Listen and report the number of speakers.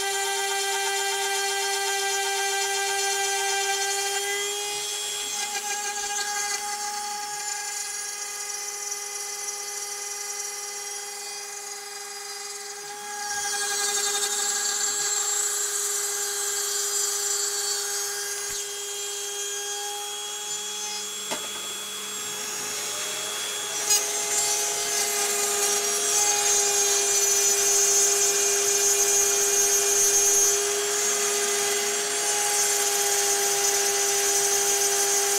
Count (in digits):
0